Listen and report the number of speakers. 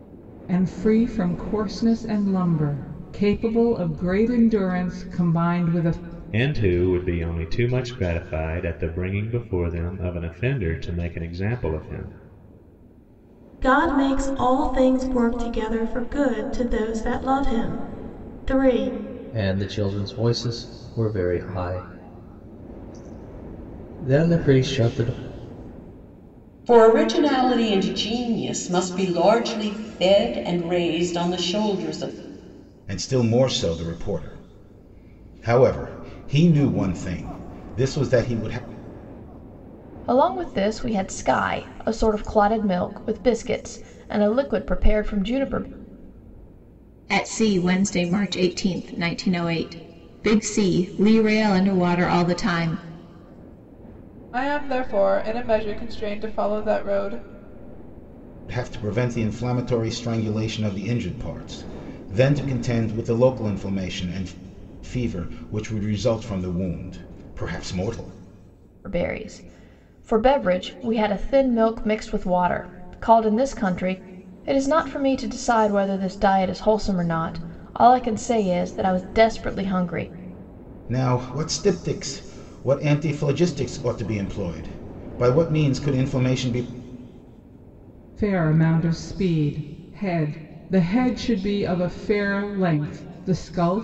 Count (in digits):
9